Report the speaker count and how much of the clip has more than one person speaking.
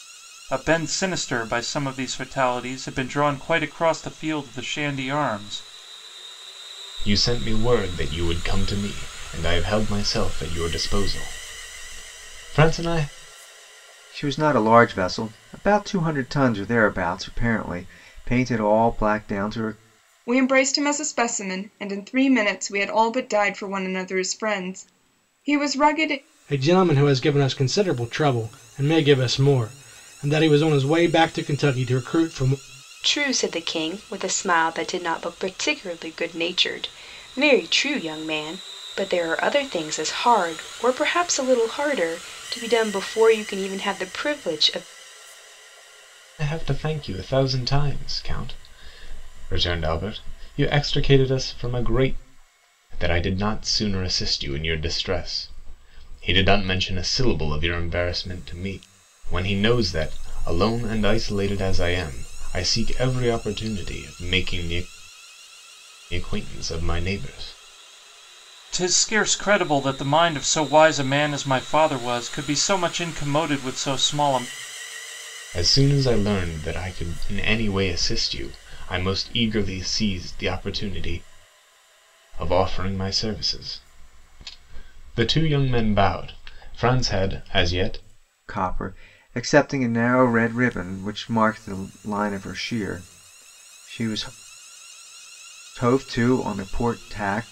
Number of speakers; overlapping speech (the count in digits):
6, no overlap